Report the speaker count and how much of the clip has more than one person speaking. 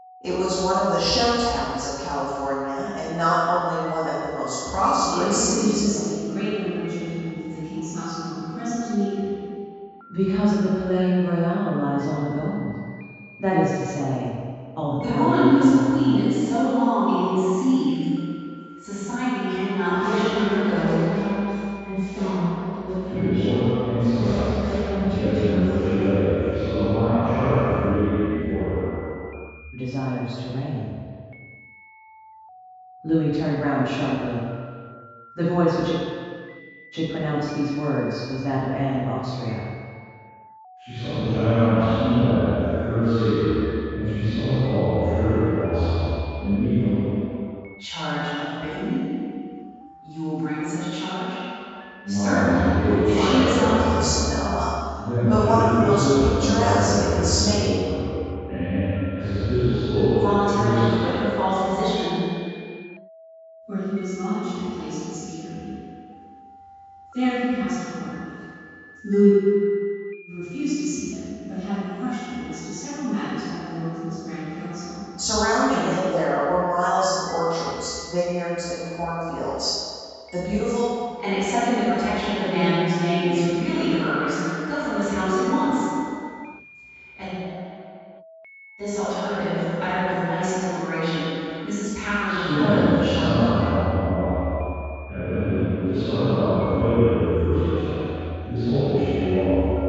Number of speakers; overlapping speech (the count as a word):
six, about 14%